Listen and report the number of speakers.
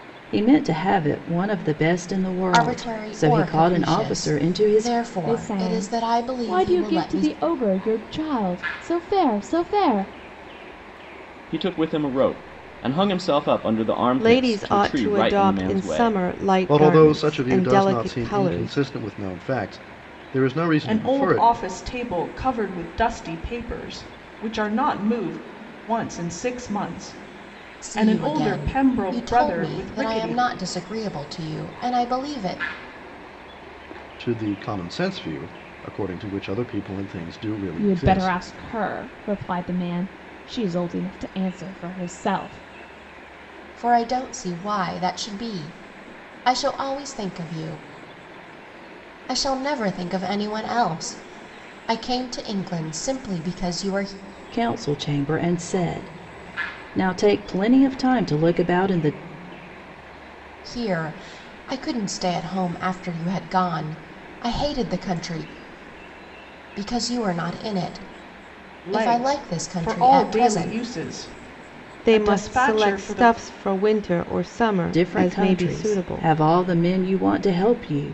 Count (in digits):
7